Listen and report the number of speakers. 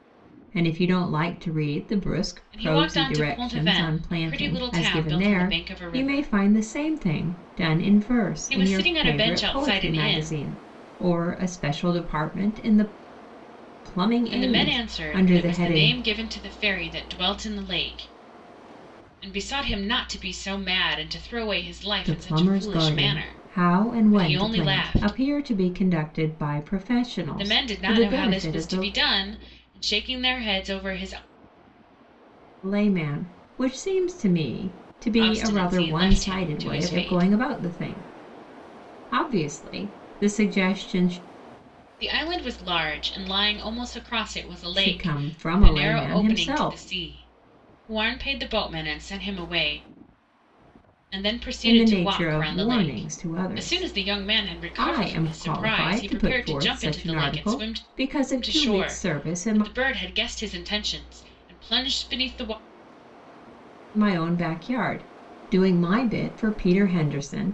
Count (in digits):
2